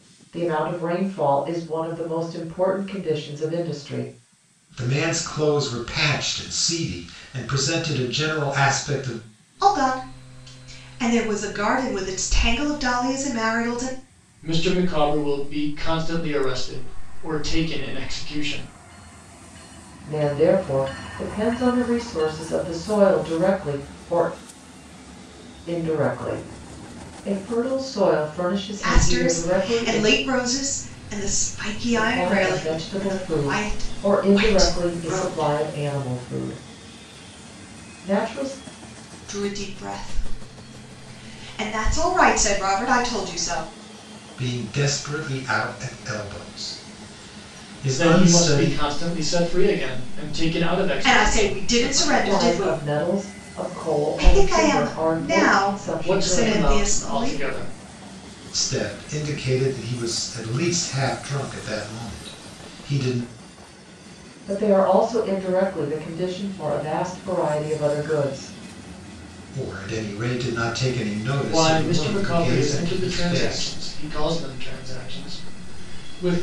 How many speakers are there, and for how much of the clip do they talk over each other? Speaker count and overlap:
4, about 17%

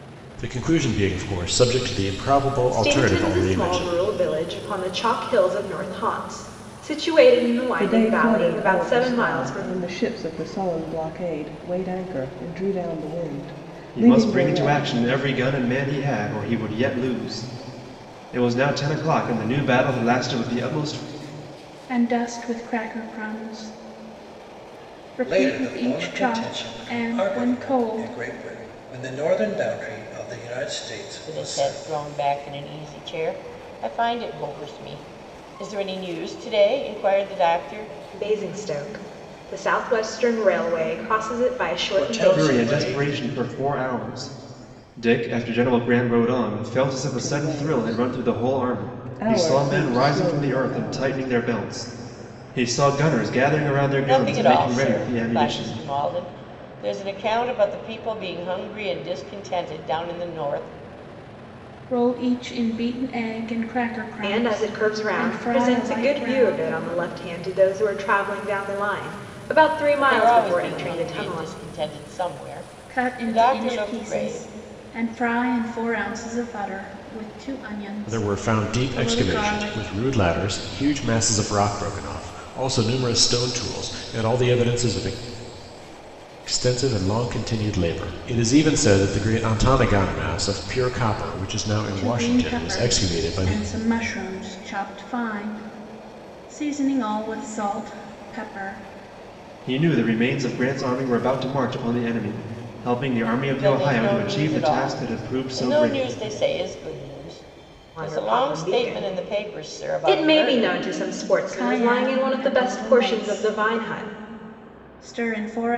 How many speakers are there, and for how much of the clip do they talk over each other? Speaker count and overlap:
7, about 28%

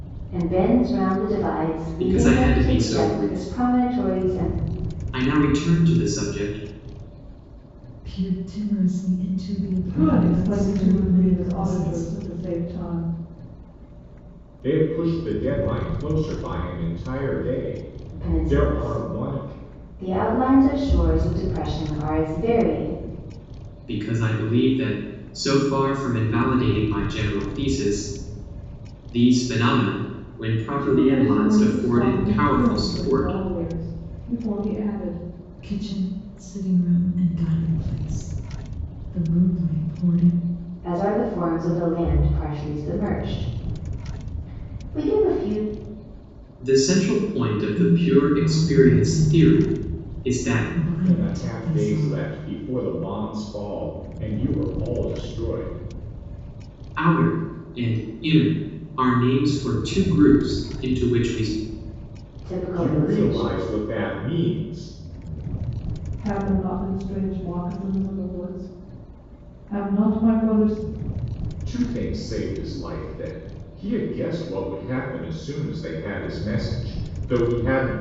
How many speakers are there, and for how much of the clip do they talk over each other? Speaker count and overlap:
5, about 18%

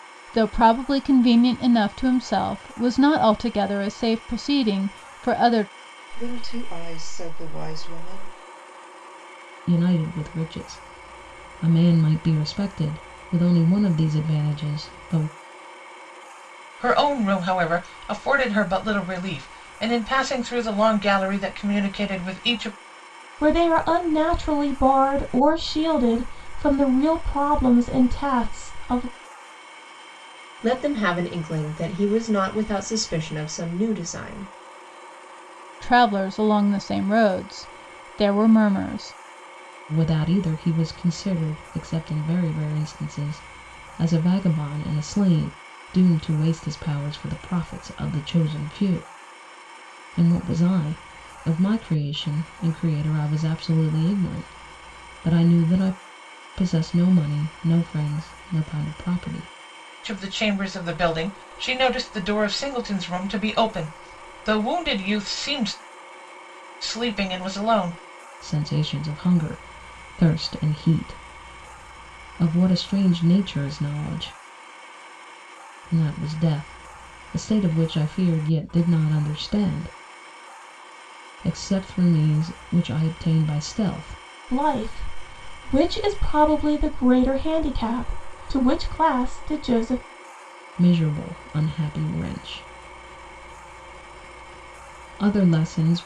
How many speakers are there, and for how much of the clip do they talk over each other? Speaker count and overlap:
6, no overlap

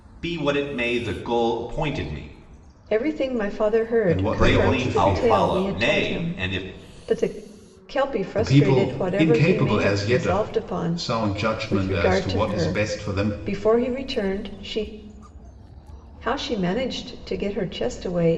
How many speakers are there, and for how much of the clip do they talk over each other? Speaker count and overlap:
3, about 40%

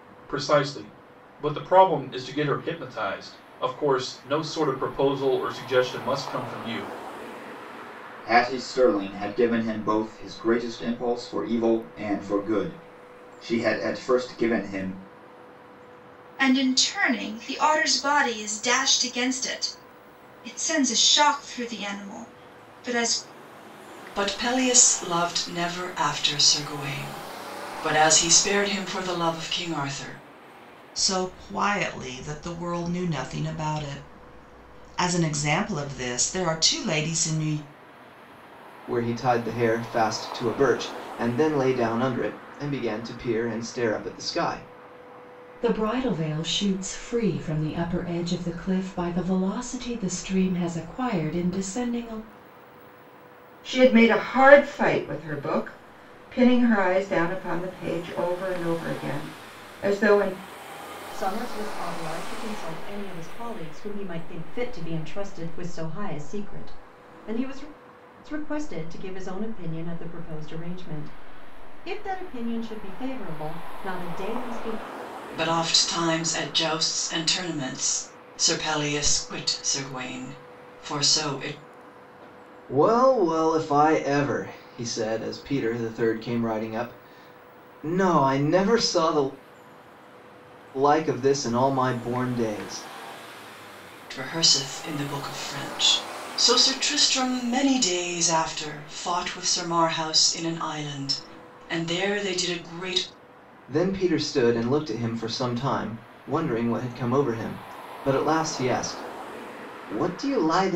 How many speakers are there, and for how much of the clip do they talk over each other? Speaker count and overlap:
9, no overlap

